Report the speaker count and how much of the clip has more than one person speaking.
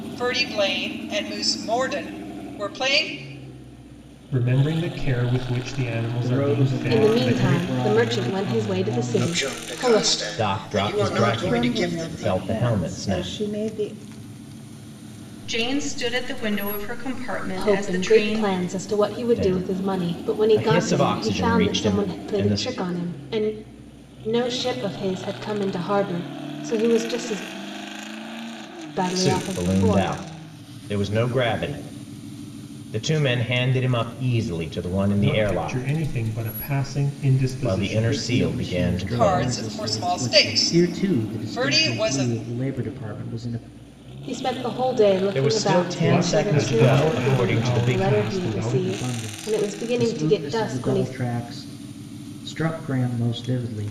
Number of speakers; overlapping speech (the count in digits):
8, about 44%